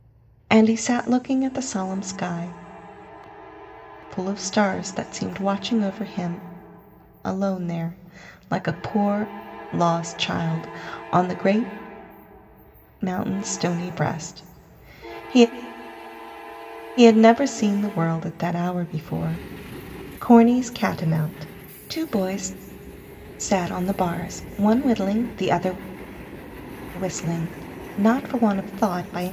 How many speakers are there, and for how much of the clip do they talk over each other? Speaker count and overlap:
1, no overlap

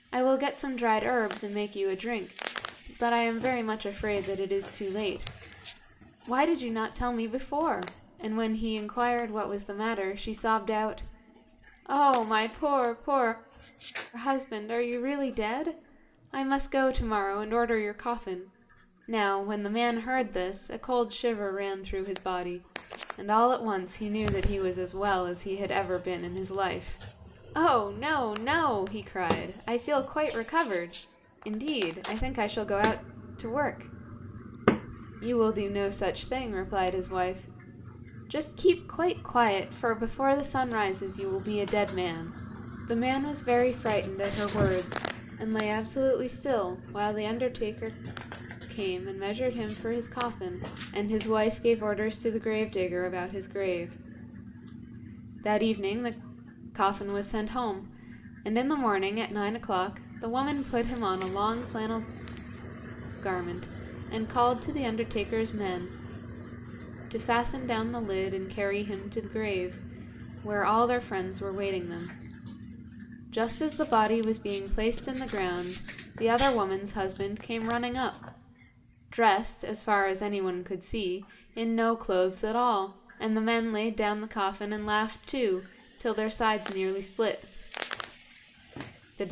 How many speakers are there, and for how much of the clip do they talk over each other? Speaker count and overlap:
1, no overlap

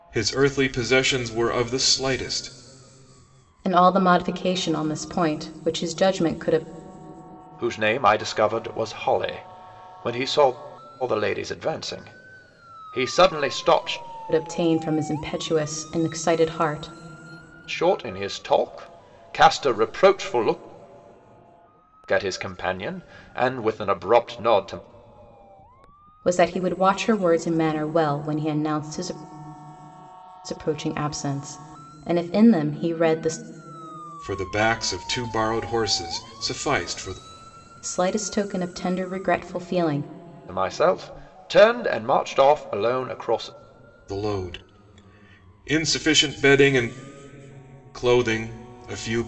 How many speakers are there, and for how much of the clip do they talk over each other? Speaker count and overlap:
3, no overlap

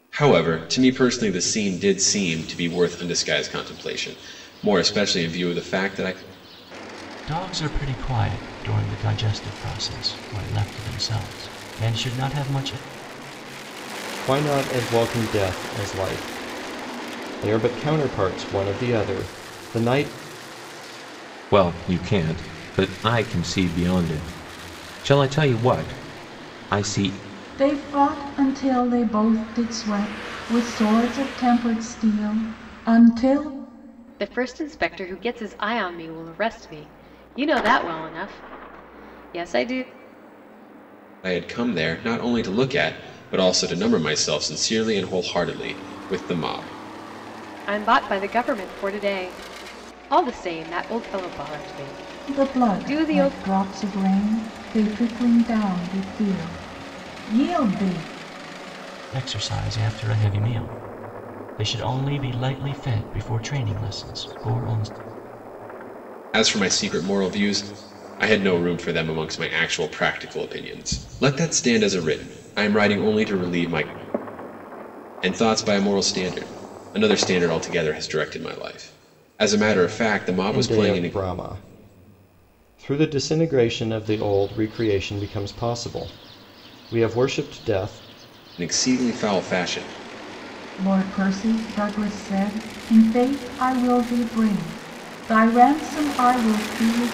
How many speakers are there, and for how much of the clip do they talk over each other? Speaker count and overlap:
6, about 2%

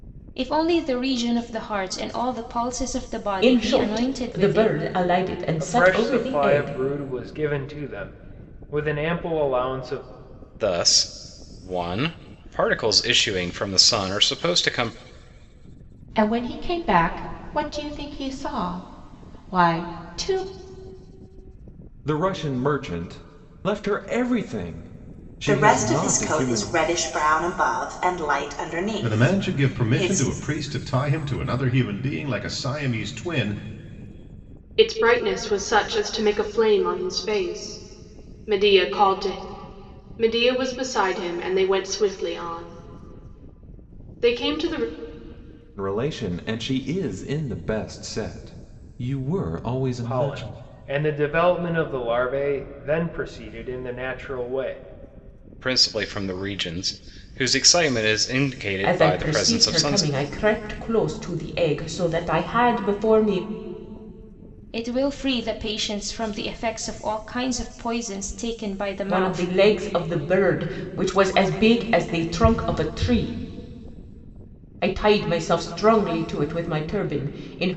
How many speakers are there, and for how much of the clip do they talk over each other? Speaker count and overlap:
9, about 10%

